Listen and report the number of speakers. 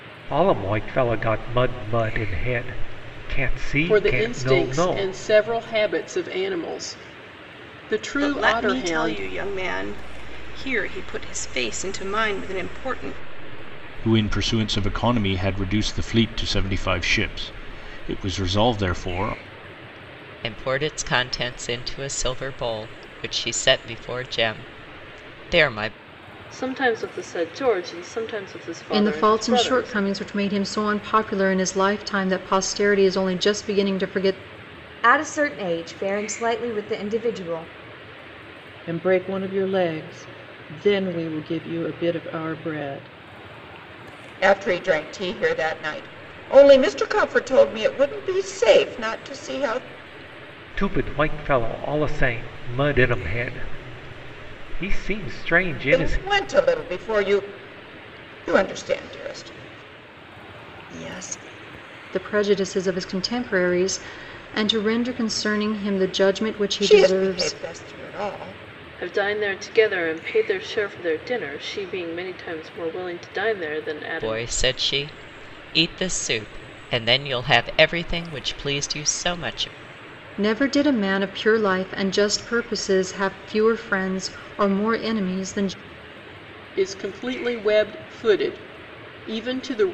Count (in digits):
10